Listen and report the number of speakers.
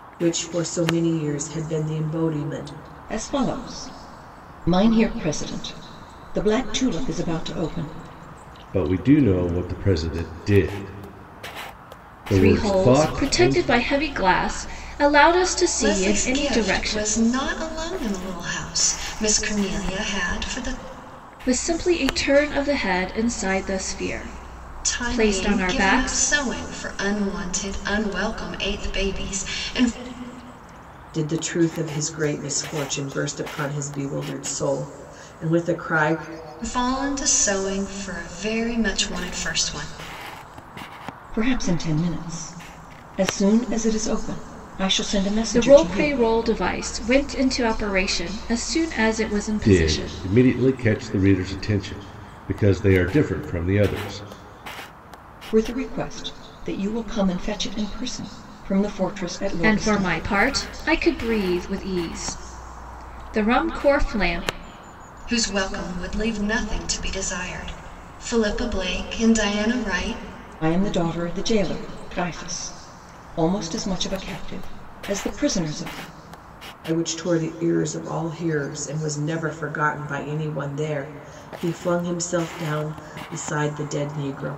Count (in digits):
5